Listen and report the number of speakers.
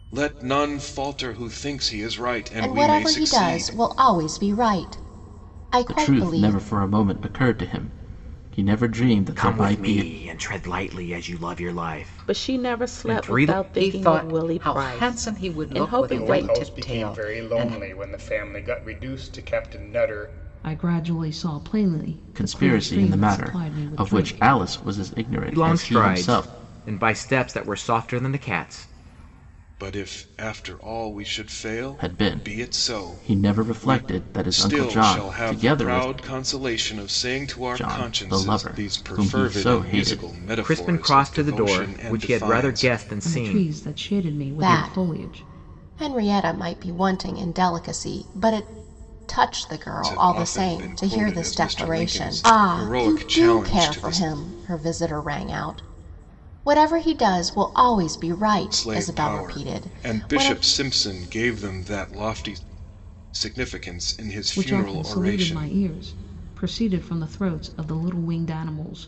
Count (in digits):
8